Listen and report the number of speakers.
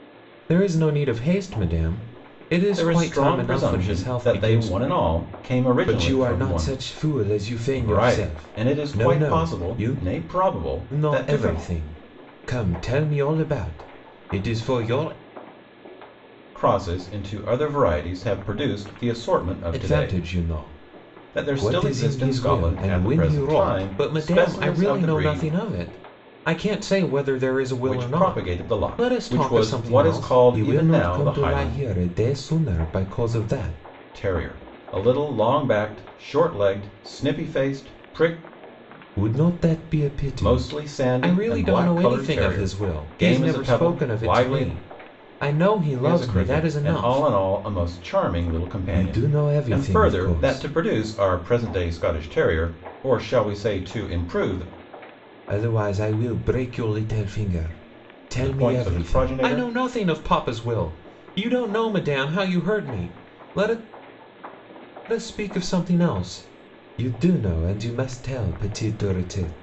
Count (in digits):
2